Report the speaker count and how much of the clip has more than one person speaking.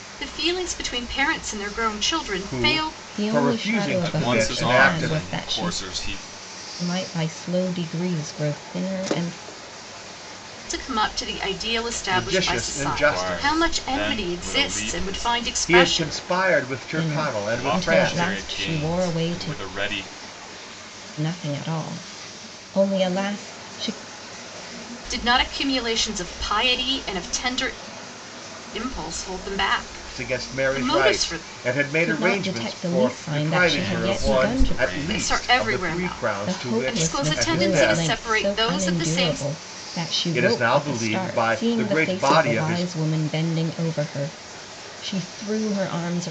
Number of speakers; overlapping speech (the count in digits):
4, about 46%